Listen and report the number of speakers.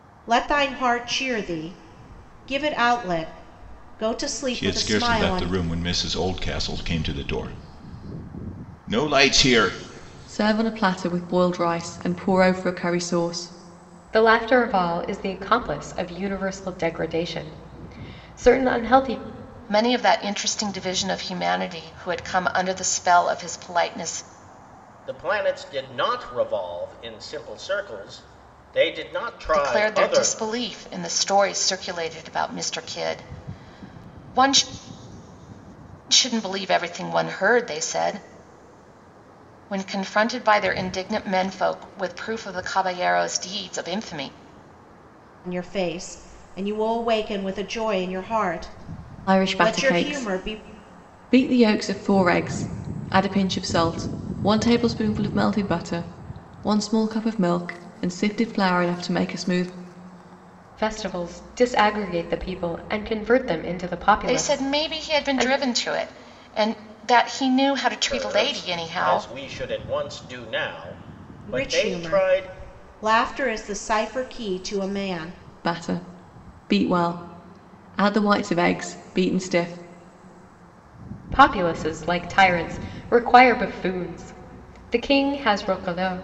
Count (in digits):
6